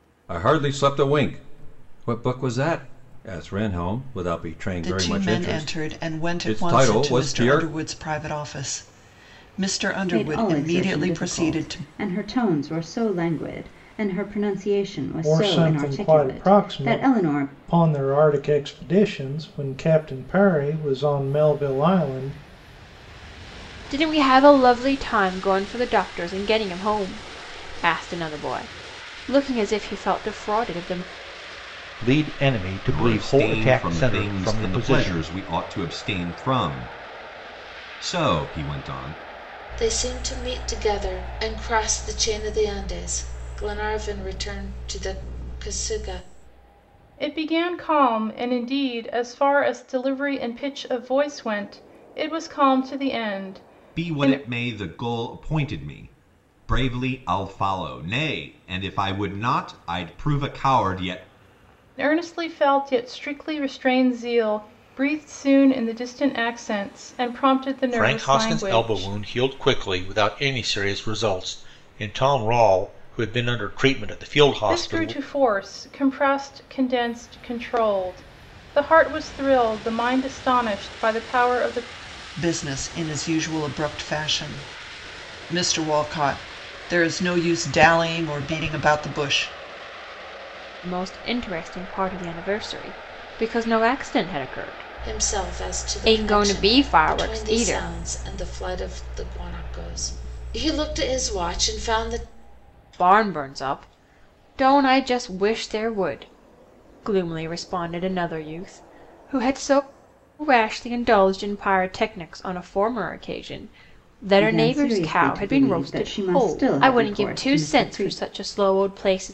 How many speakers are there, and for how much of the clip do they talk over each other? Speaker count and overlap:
9, about 16%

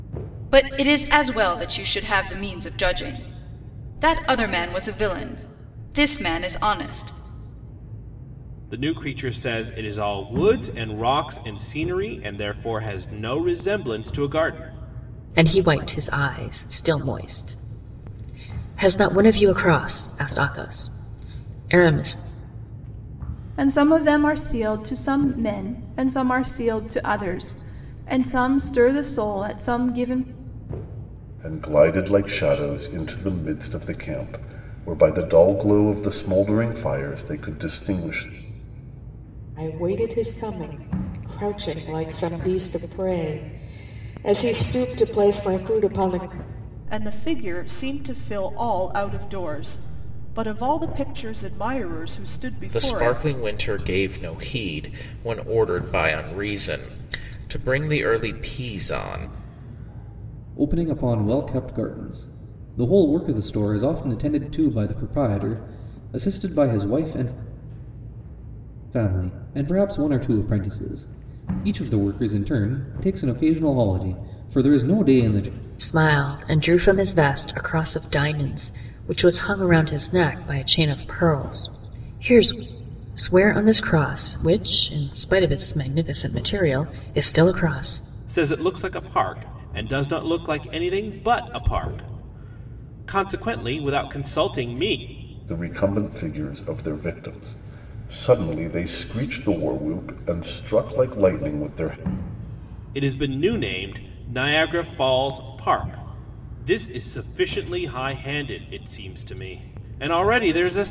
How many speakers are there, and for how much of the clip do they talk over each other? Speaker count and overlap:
9, about 1%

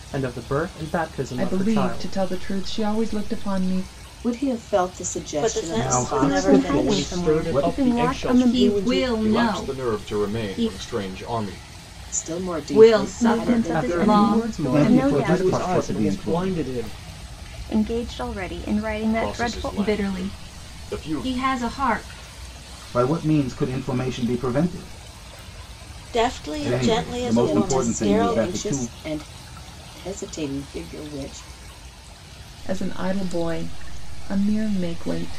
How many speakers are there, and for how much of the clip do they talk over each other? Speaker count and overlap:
9, about 41%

